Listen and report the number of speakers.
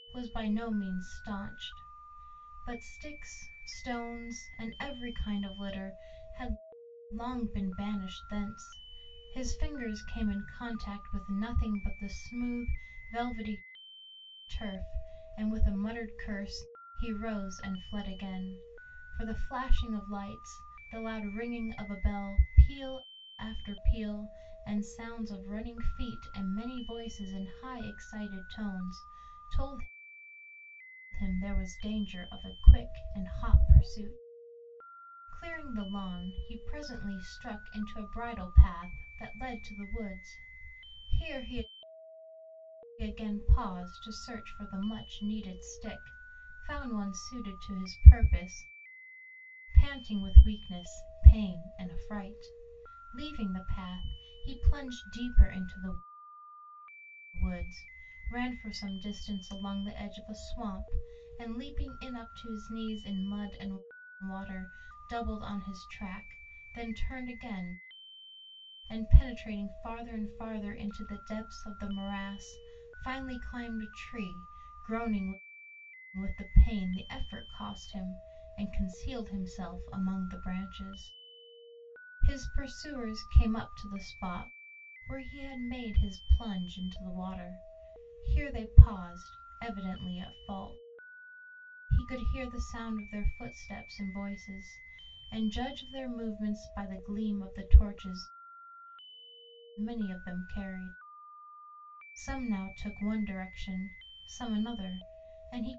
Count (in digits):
1